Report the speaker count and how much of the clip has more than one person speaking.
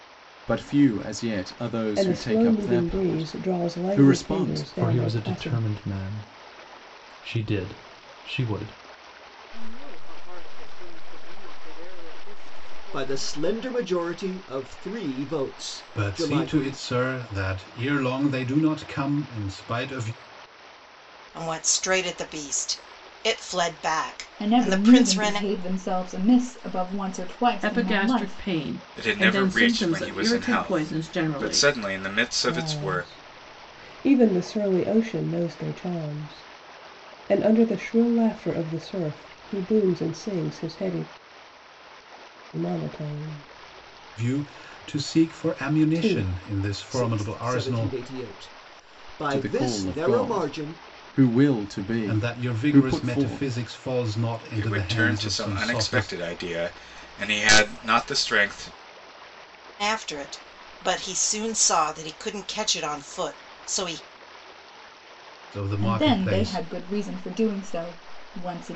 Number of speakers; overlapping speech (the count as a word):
ten, about 28%